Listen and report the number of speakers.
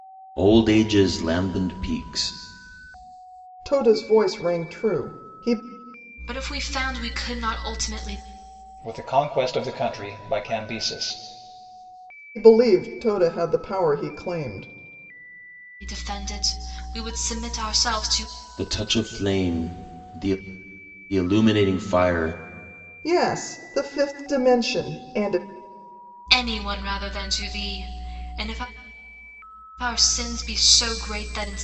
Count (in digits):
4